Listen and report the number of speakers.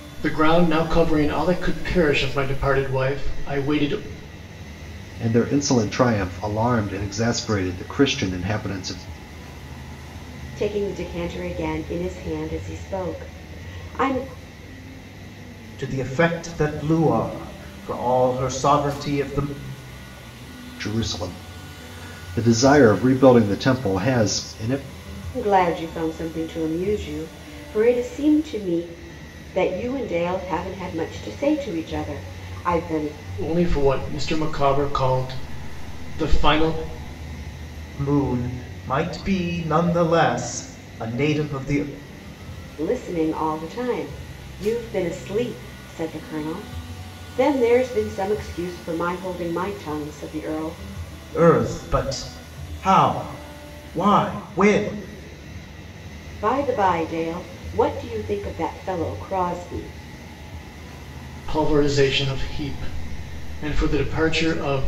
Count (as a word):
four